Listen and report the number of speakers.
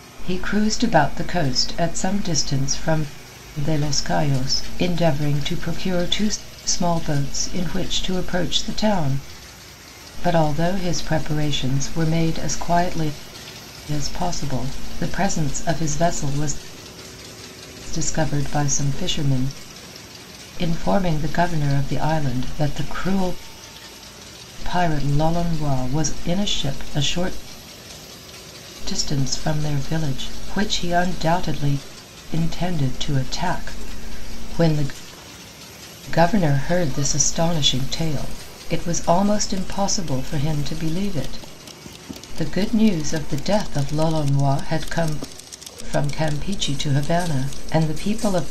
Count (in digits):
1